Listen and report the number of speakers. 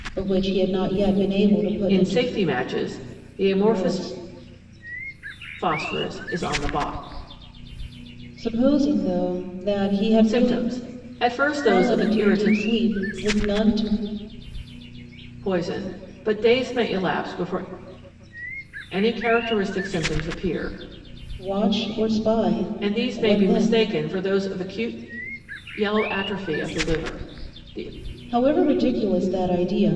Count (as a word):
two